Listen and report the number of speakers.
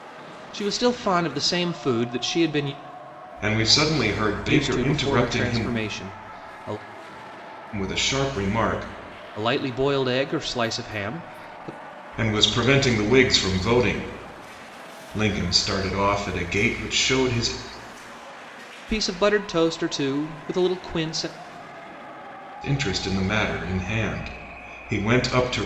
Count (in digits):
2